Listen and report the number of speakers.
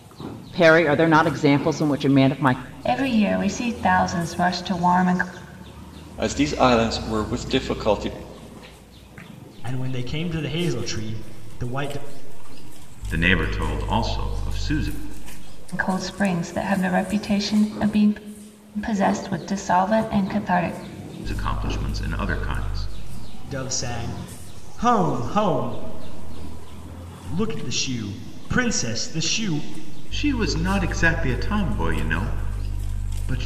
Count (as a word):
five